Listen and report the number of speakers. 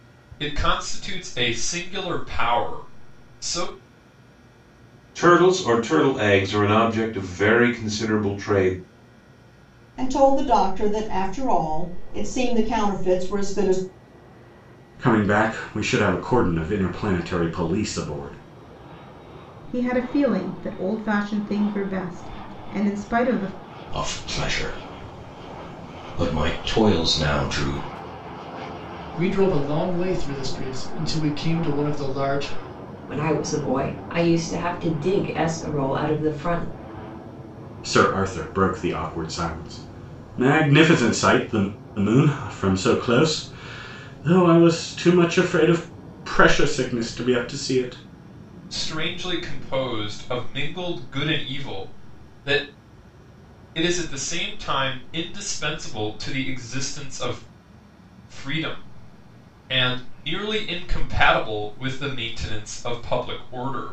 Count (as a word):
eight